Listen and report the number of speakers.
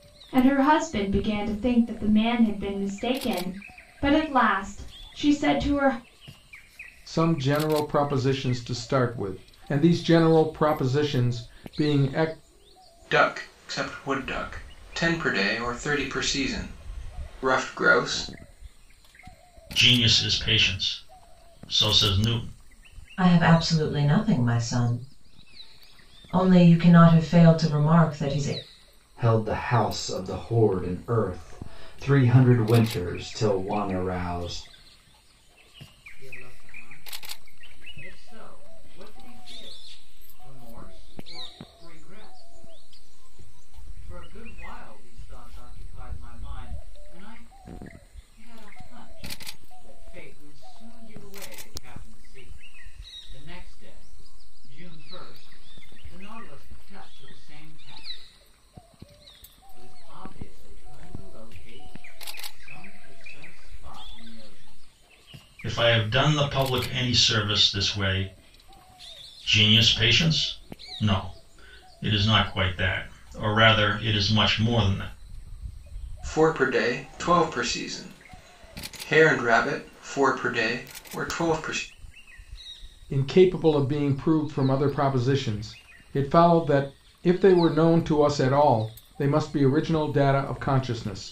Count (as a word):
seven